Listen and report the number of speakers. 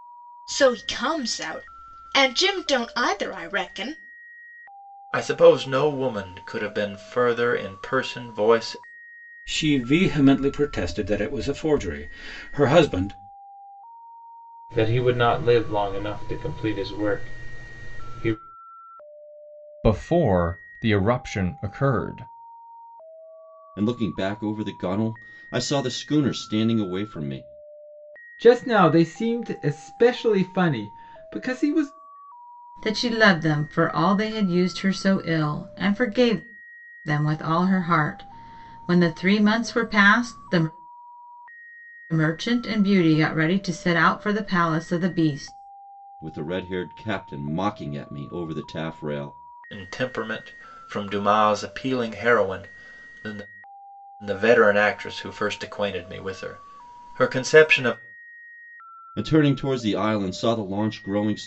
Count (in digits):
8